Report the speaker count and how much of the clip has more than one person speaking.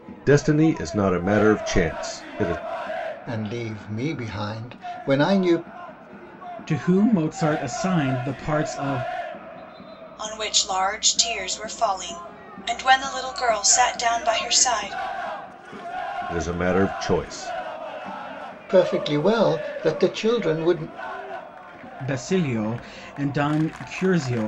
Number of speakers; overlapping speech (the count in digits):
4, no overlap